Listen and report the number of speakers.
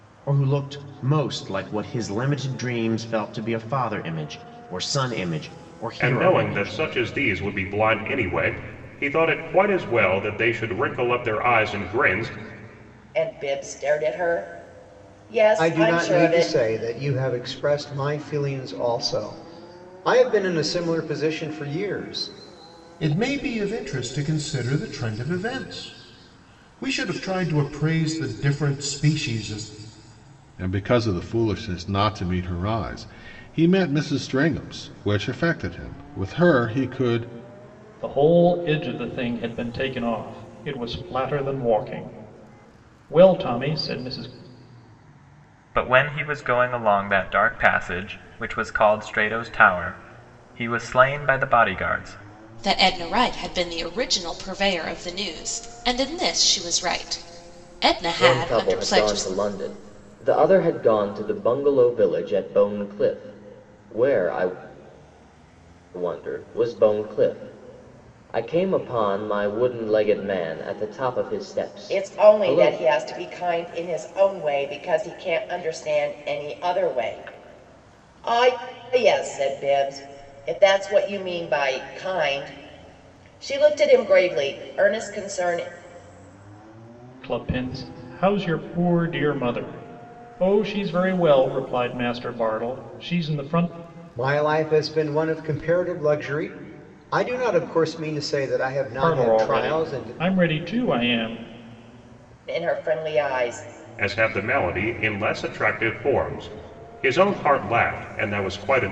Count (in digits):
10